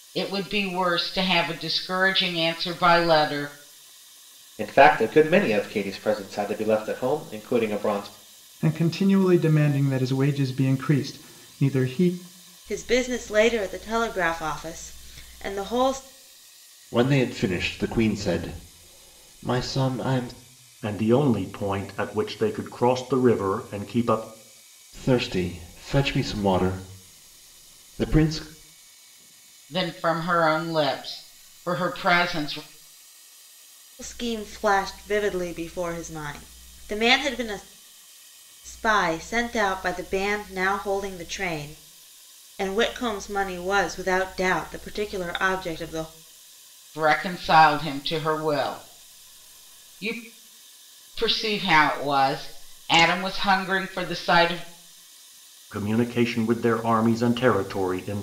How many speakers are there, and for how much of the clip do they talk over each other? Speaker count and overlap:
6, no overlap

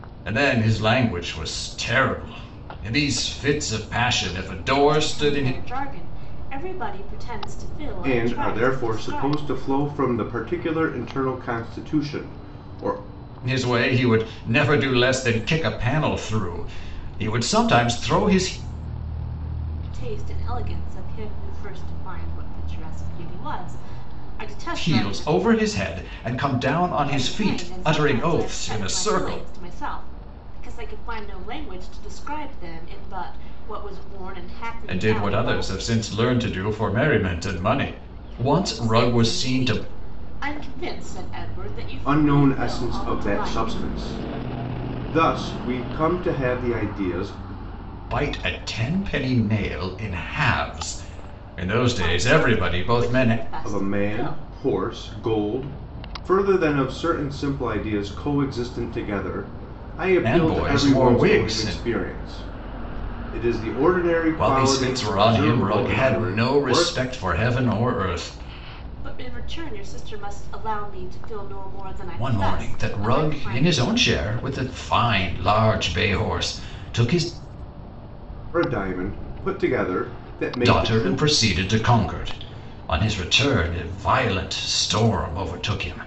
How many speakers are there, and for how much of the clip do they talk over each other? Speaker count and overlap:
3, about 21%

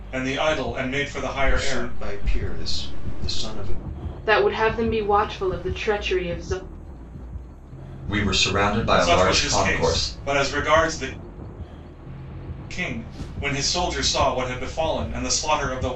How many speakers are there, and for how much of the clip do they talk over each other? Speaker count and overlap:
4, about 11%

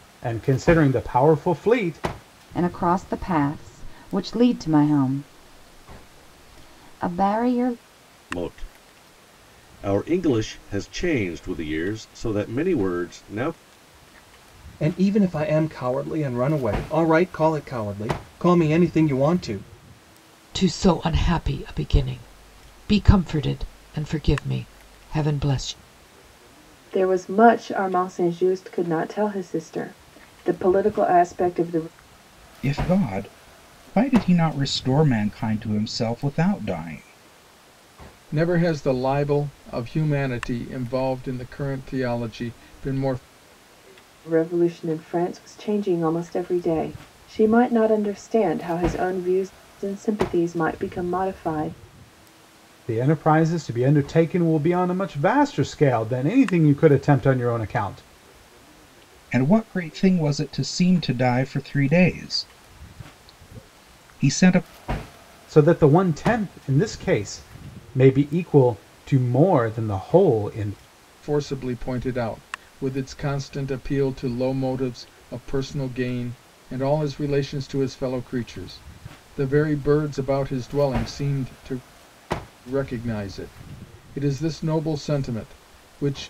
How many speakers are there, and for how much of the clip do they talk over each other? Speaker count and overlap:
8, no overlap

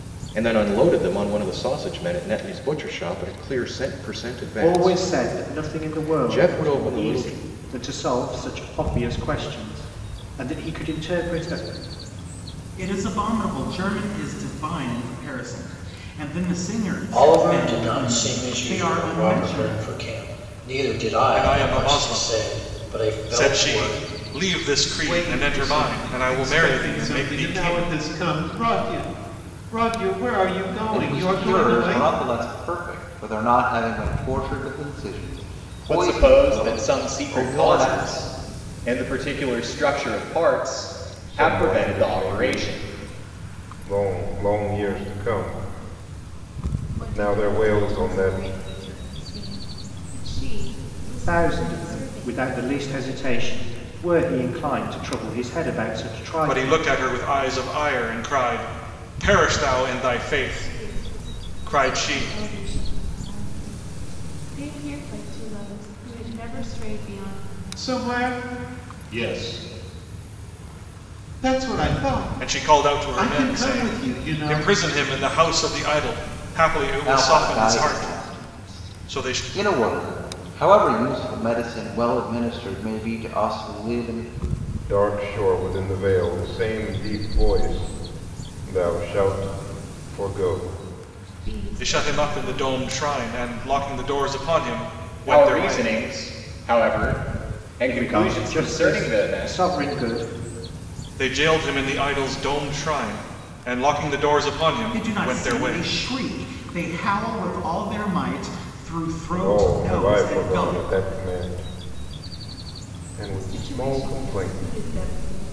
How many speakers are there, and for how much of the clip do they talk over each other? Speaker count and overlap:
10, about 30%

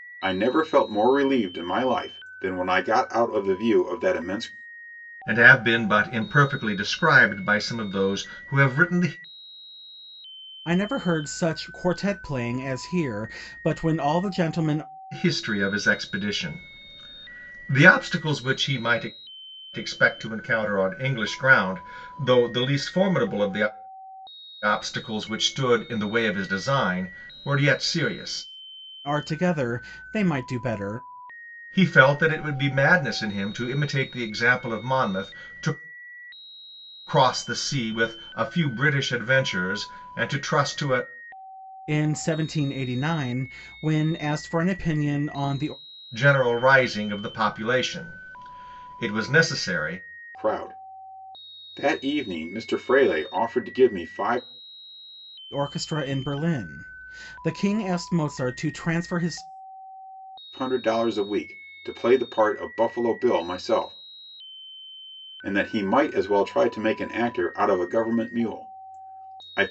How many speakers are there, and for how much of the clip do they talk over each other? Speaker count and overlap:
3, no overlap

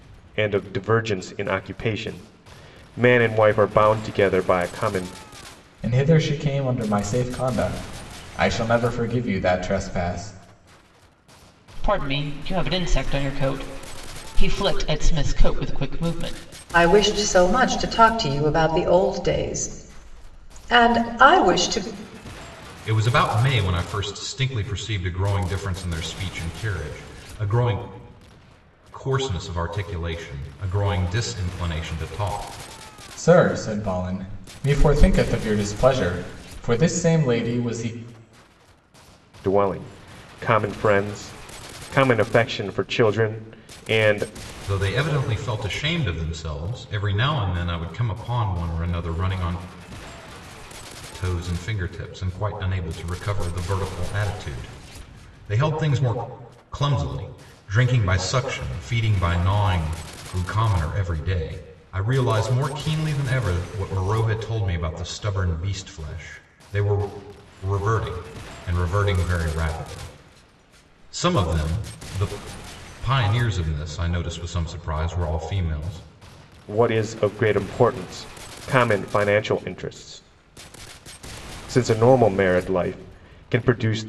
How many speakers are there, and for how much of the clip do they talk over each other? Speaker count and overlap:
5, no overlap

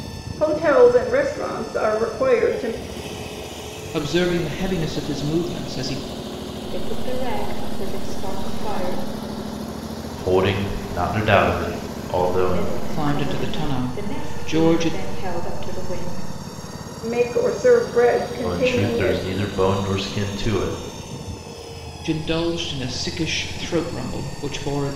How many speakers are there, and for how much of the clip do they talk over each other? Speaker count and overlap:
4, about 13%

